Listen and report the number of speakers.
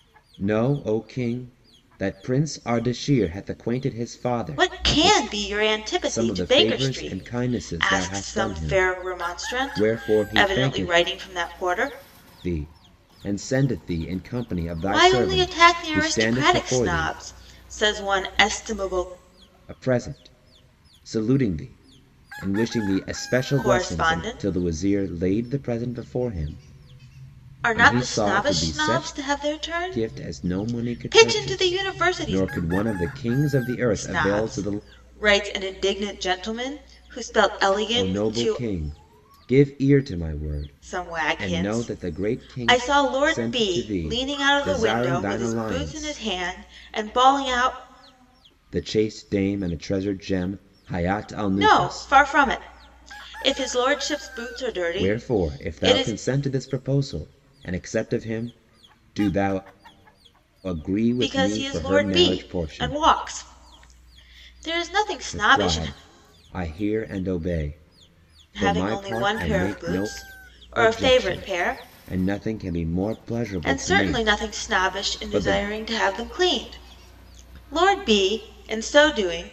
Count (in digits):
2